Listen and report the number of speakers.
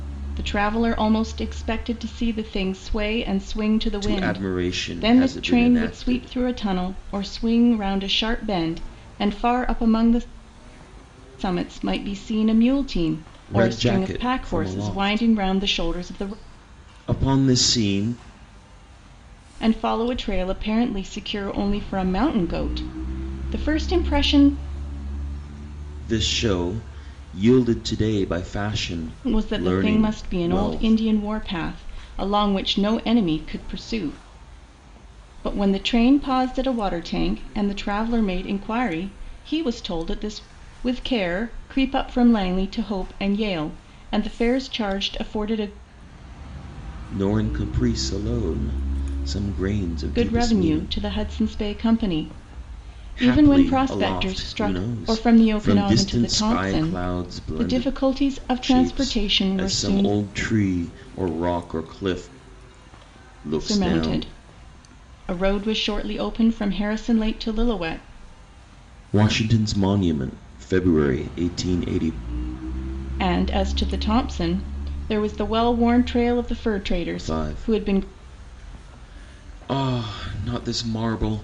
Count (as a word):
two